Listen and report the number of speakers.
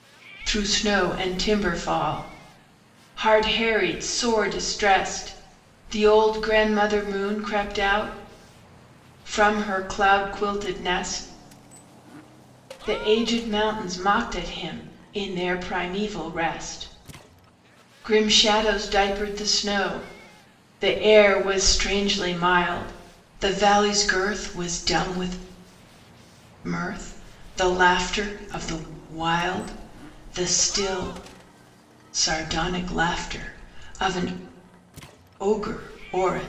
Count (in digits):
1